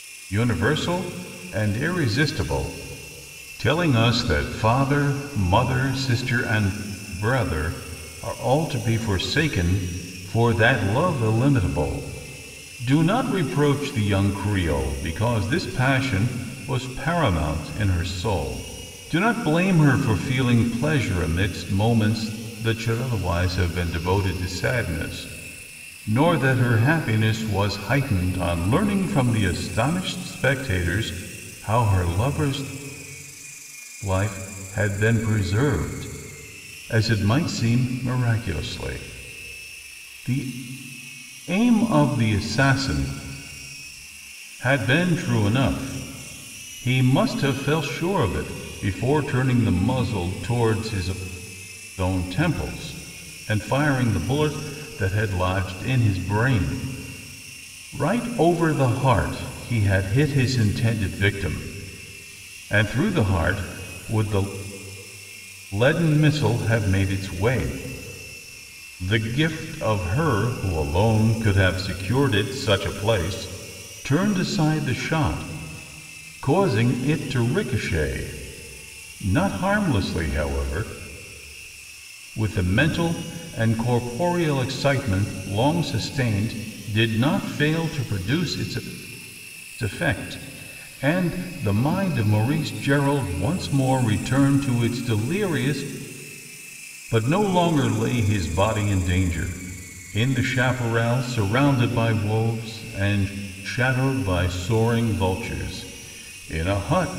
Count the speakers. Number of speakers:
1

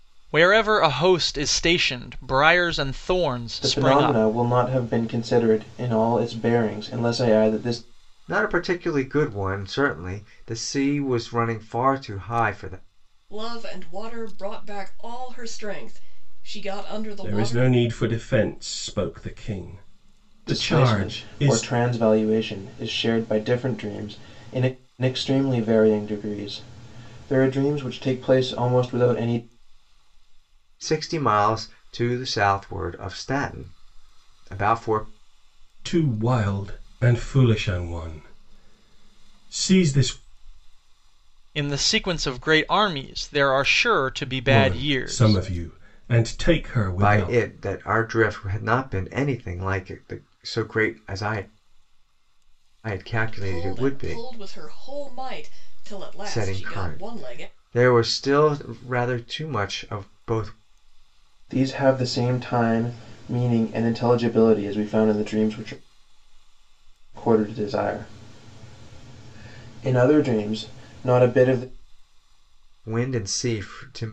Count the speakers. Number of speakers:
5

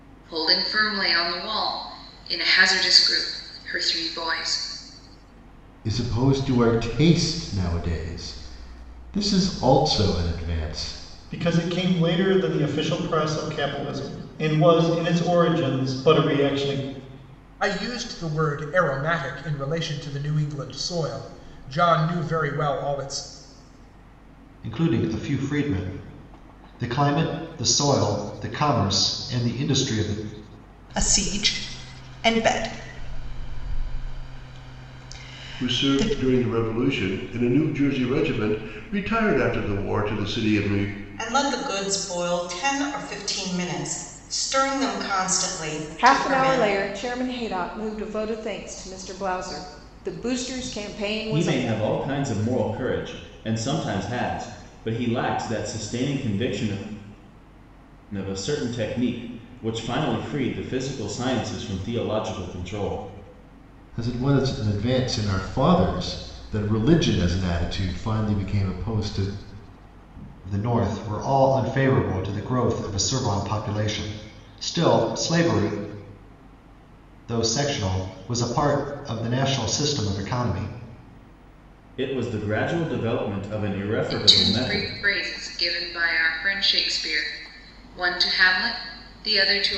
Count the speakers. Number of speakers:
10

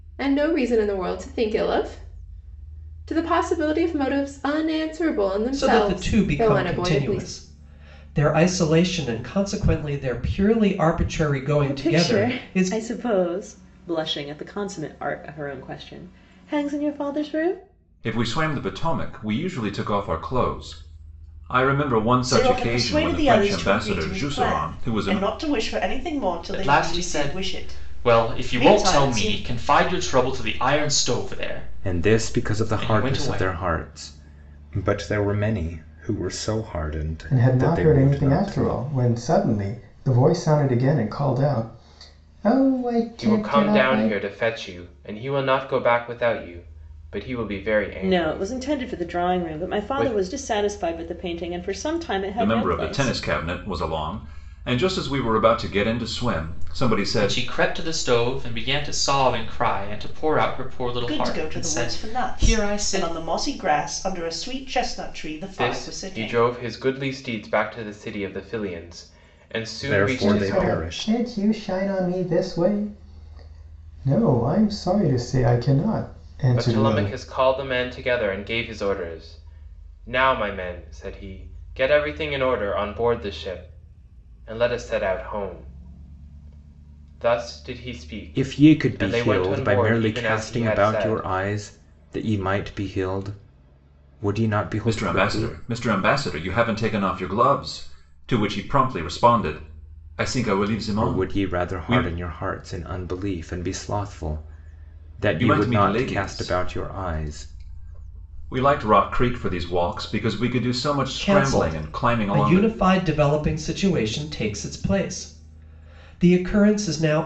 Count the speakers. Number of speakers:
9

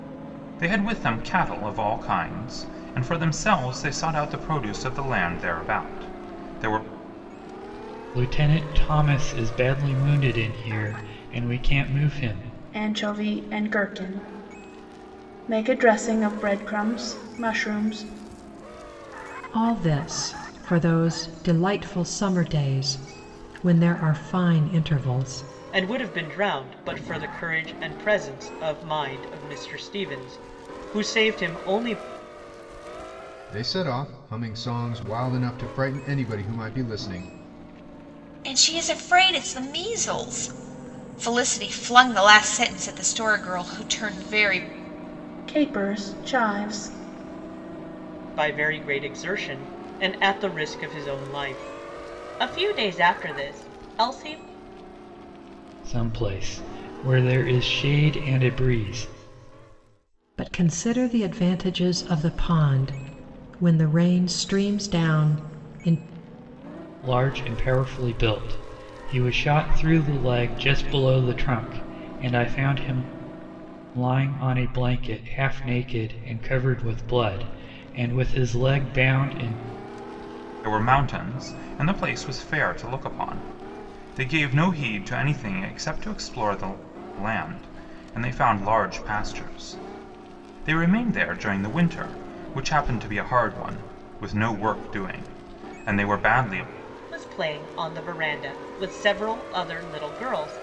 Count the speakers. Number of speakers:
7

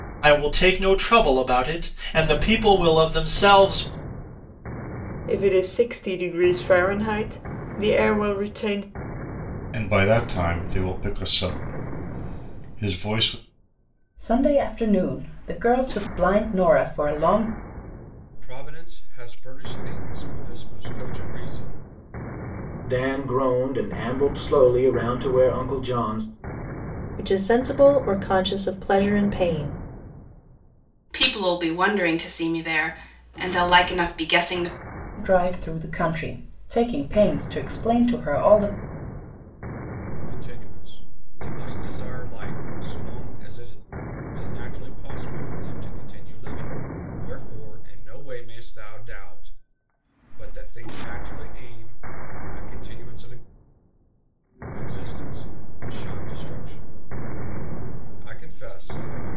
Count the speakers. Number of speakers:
8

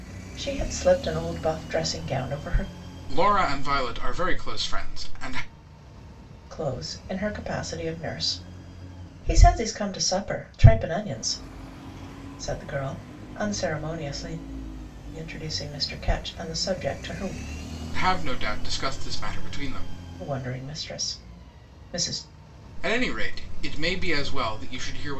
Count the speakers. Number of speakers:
2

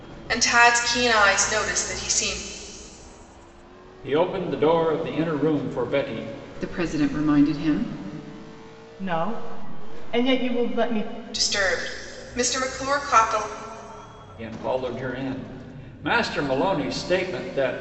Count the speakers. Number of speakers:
4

